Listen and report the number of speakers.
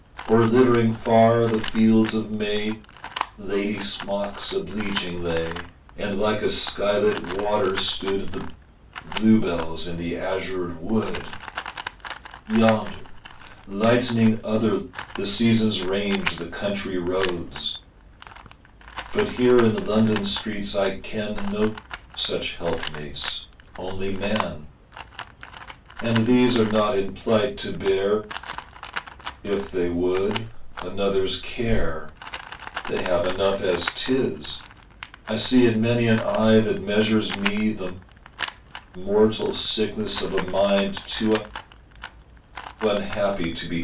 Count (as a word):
one